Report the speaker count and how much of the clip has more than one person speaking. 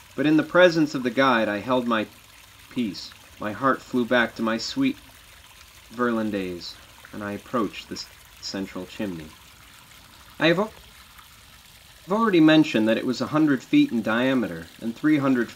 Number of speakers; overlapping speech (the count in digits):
1, no overlap